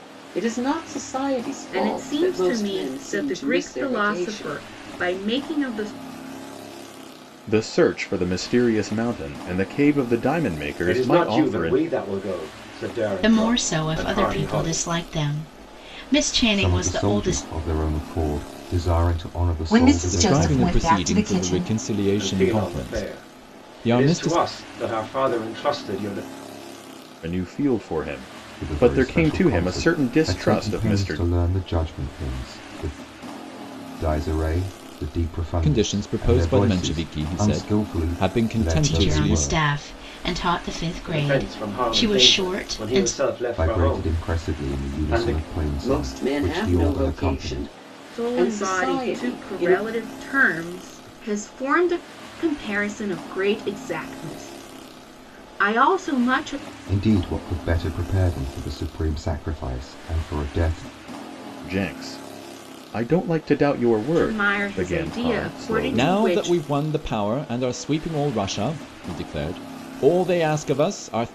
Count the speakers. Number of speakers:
8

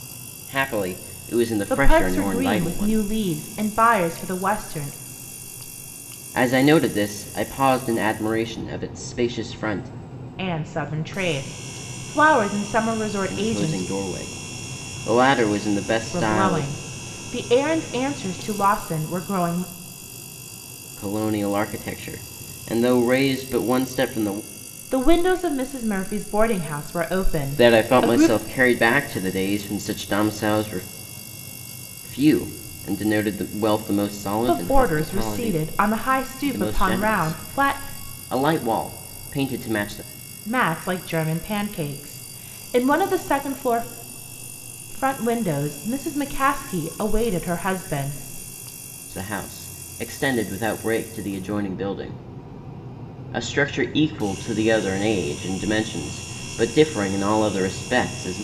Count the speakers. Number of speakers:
2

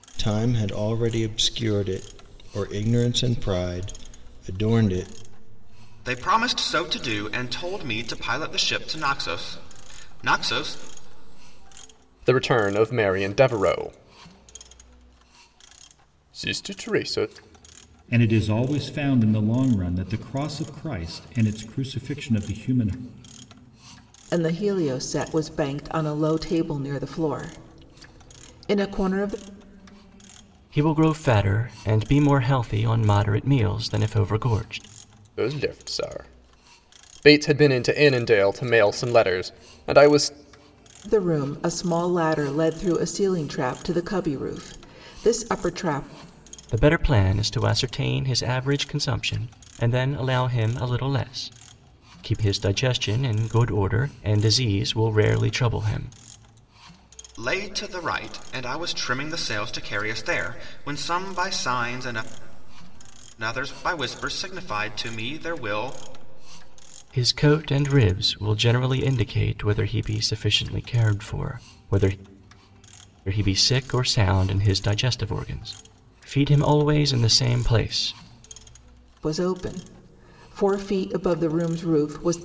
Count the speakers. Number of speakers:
6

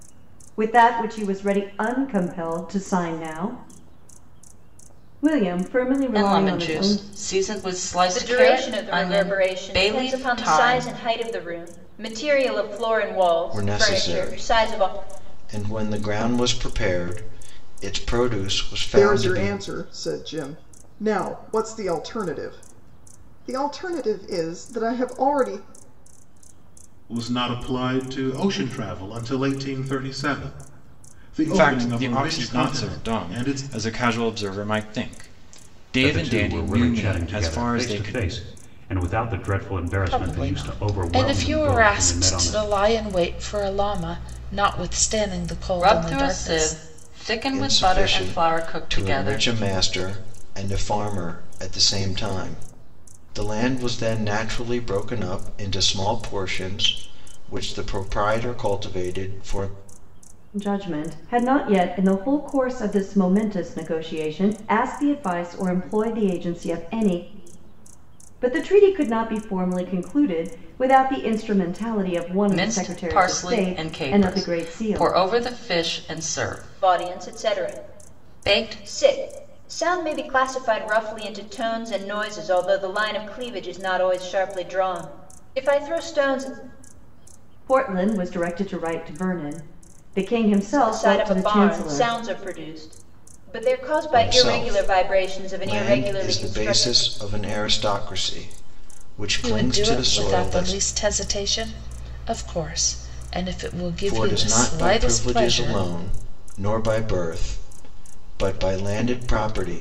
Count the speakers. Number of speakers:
9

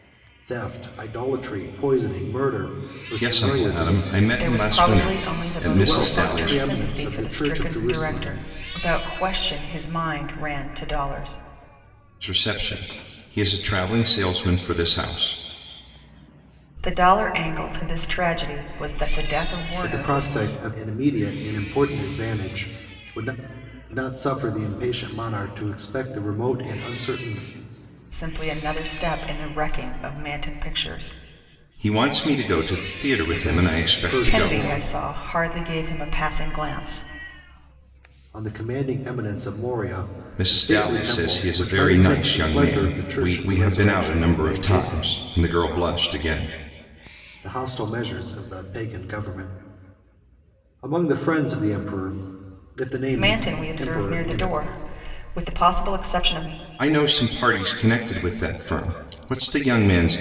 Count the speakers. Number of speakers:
3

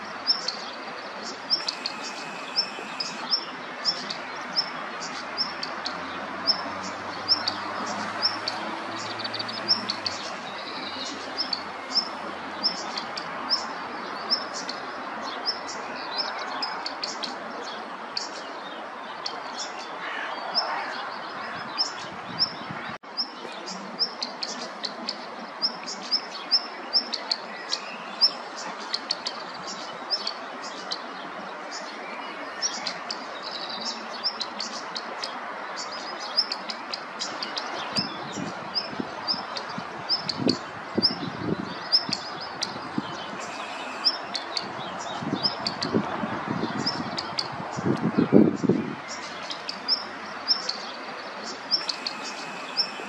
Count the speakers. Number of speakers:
0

